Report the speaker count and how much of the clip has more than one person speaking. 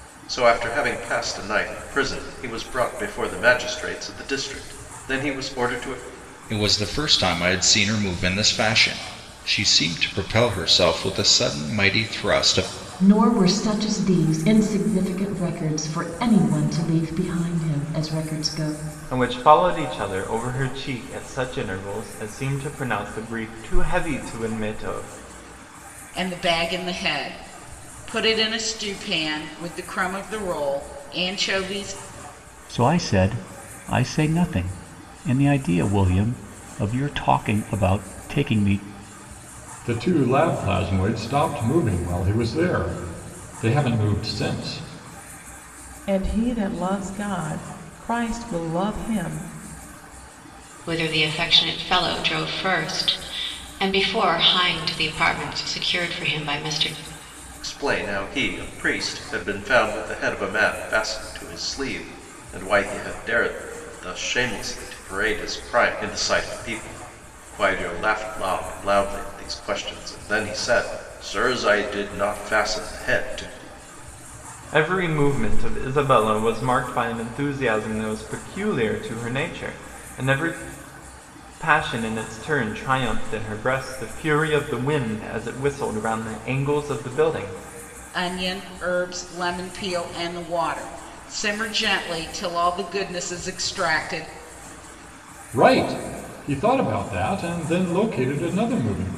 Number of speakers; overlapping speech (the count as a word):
nine, no overlap